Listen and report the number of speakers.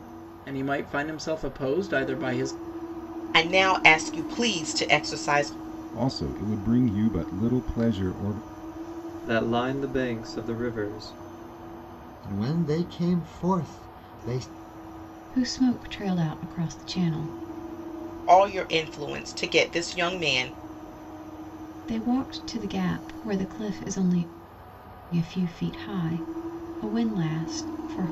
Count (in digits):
6